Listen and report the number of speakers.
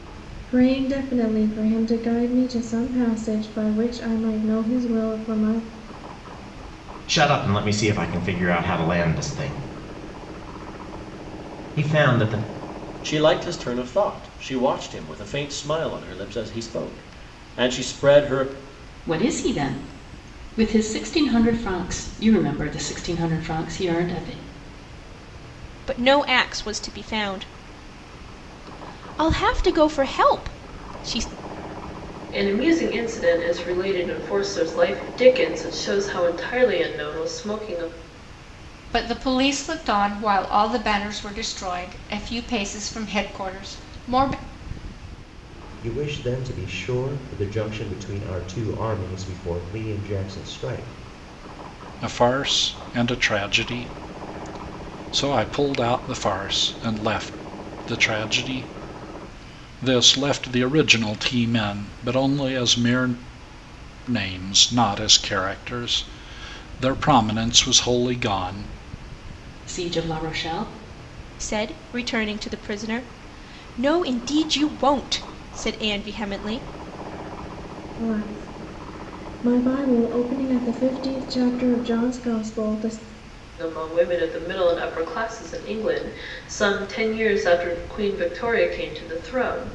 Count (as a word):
nine